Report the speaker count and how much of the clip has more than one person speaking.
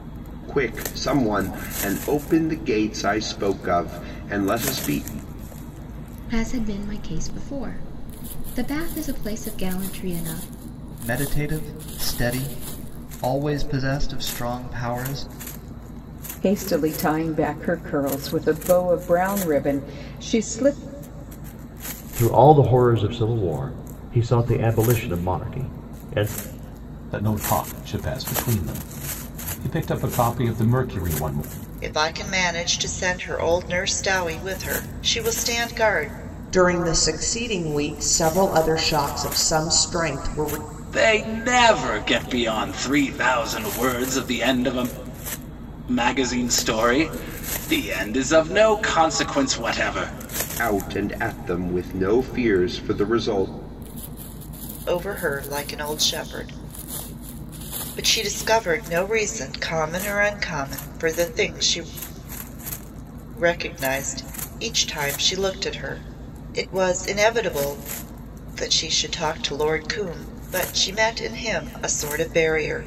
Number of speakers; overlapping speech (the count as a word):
nine, no overlap